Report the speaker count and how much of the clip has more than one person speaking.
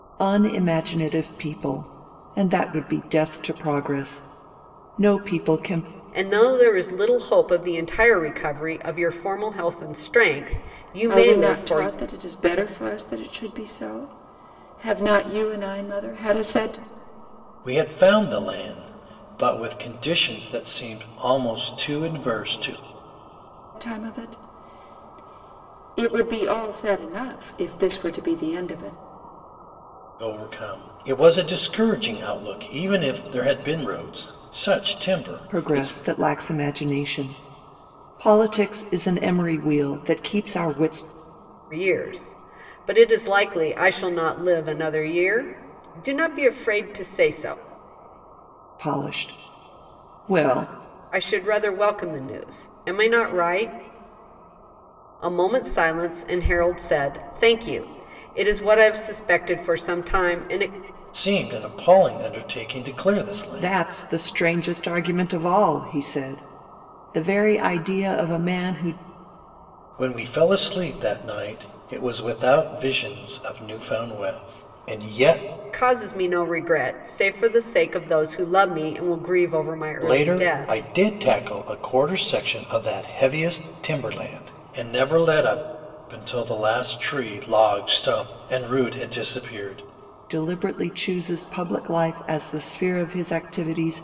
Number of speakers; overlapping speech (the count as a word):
four, about 3%